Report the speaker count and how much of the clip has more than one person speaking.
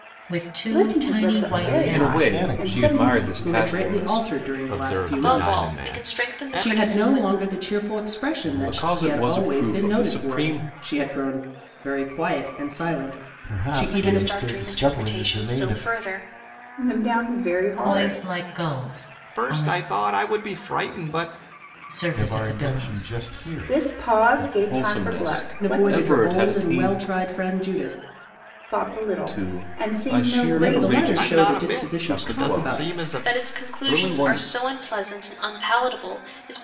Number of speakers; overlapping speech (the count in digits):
7, about 58%